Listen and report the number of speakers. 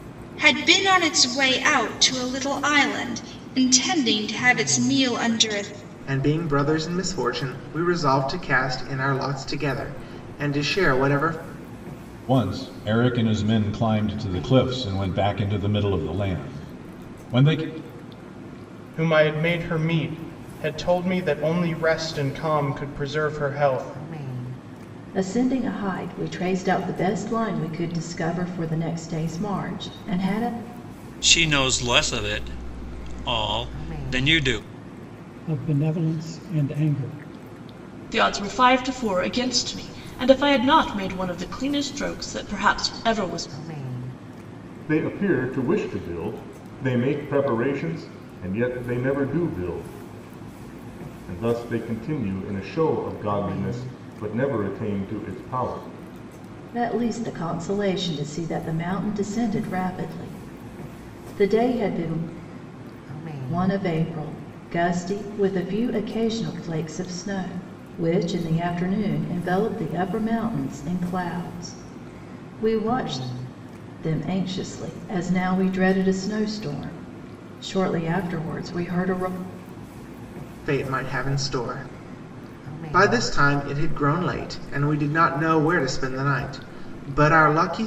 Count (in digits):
9